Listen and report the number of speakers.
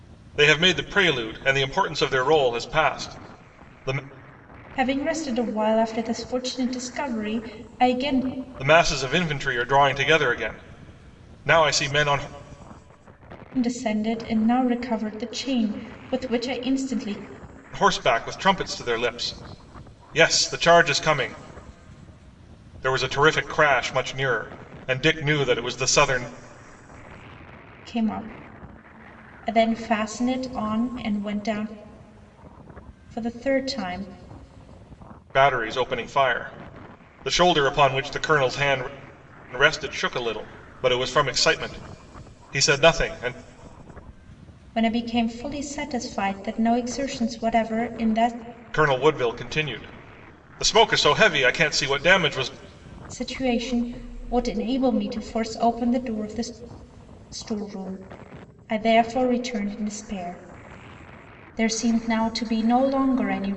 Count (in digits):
2